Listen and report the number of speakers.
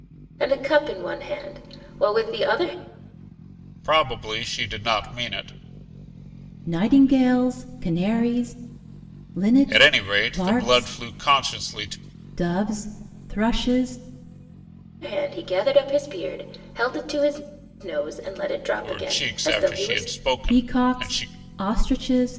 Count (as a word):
three